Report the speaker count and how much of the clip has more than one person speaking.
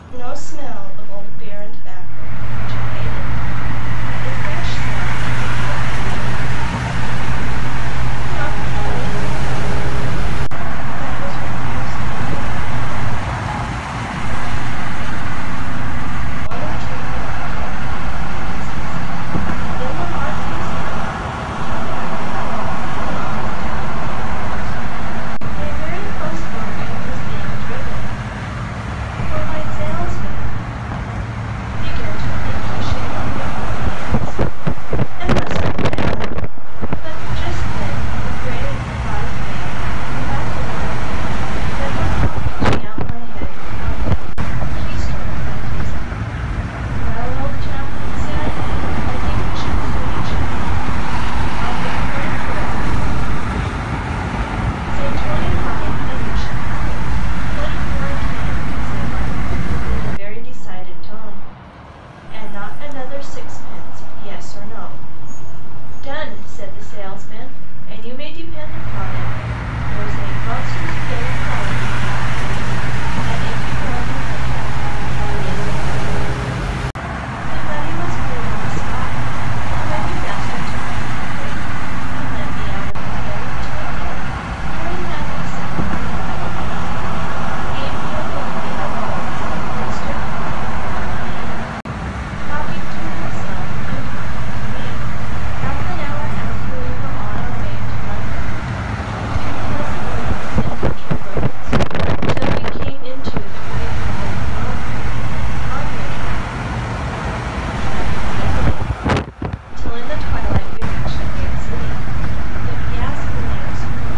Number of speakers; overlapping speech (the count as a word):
one, no overlap